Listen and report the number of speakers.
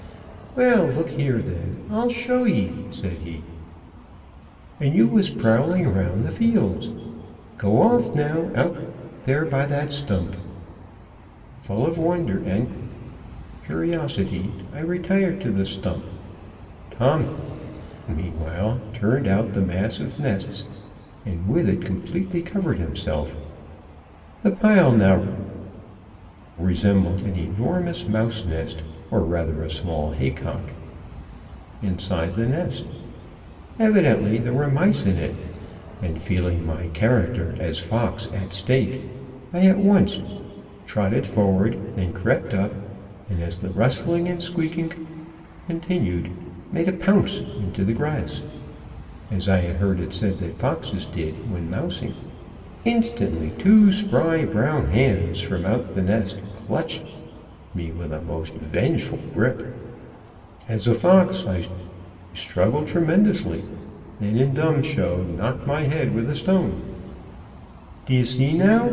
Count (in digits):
1